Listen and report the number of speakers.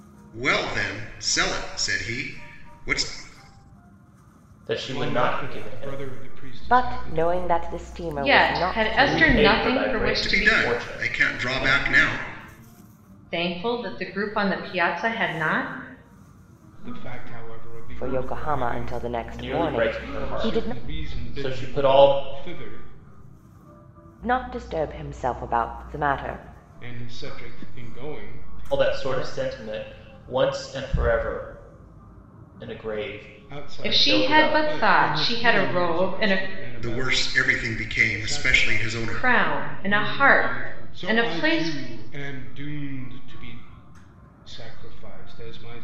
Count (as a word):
five